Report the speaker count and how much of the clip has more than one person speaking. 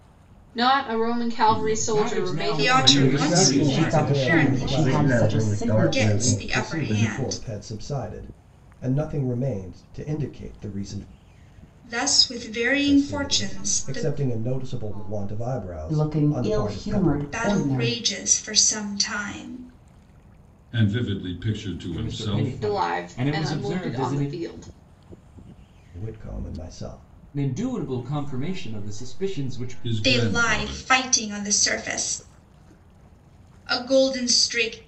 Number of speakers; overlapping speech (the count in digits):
9, about 47%